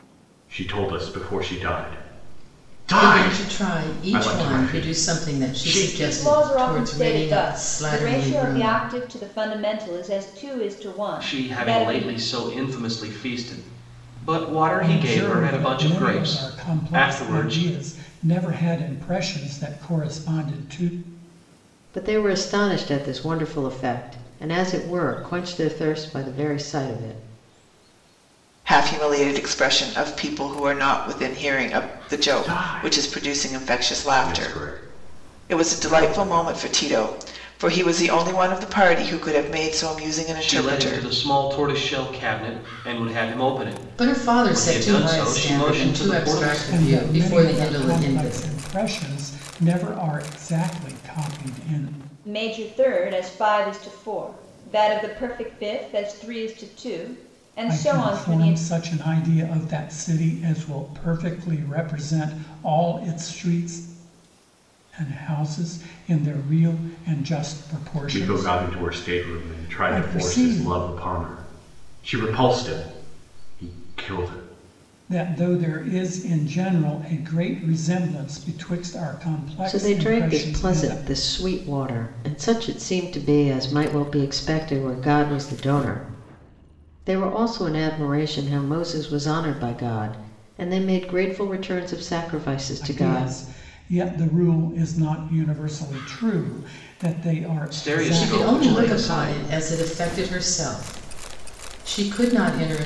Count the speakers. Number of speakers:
seven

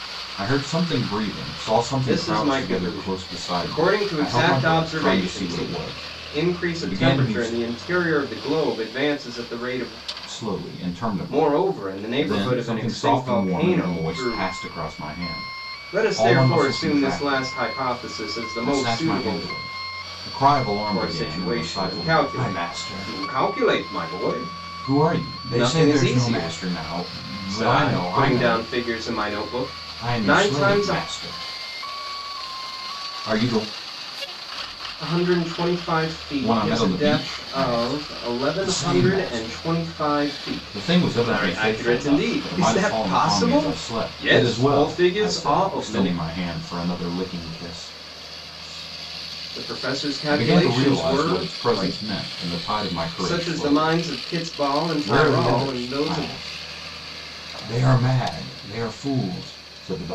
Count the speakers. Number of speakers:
two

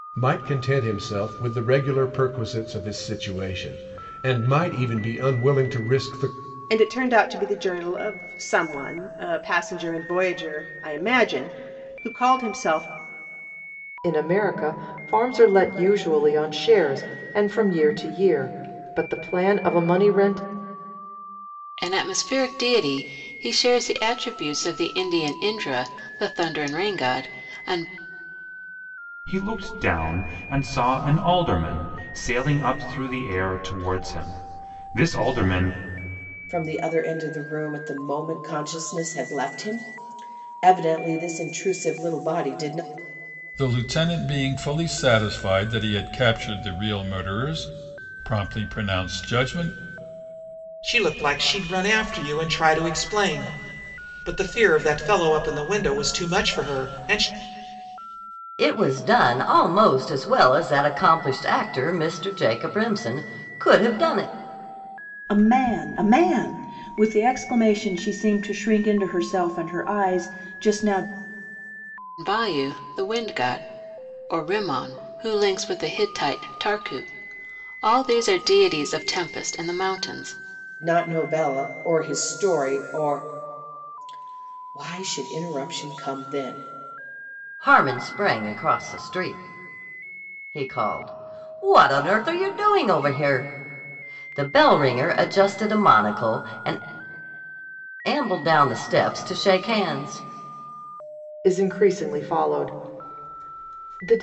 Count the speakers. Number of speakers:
ten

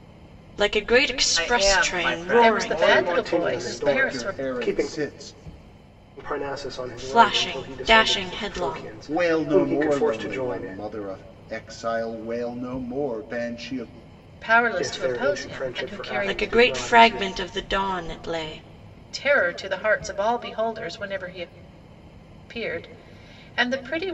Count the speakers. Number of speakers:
five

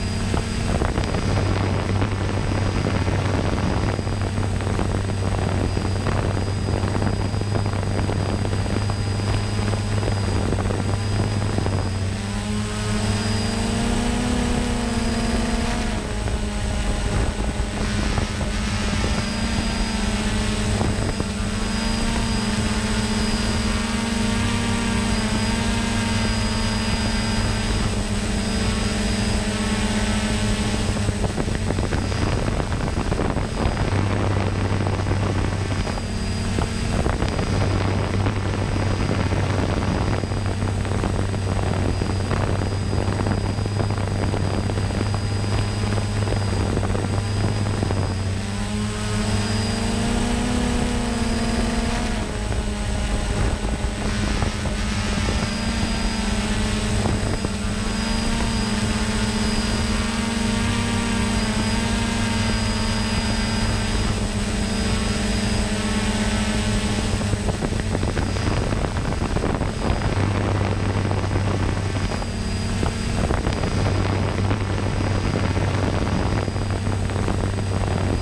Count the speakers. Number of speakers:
zero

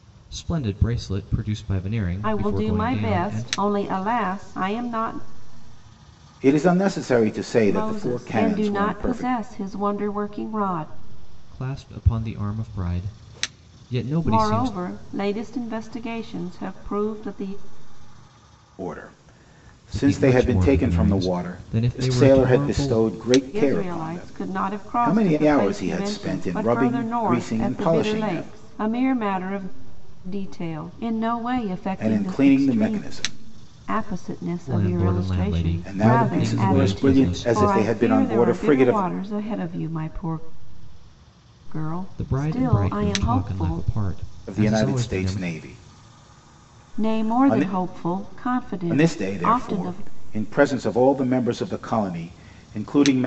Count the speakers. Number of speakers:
three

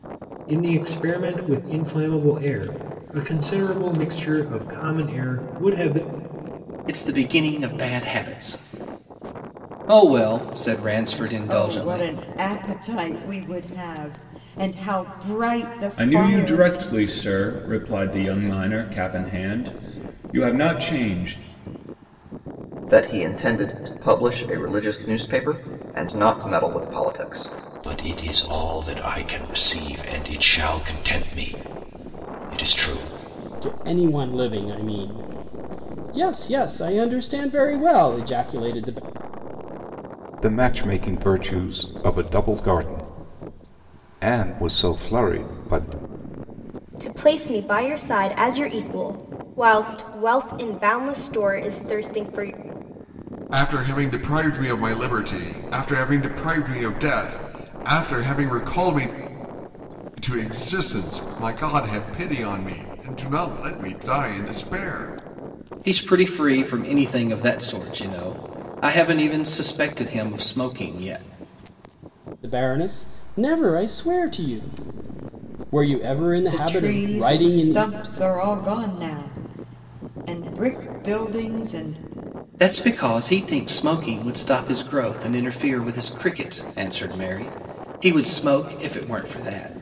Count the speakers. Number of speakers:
ten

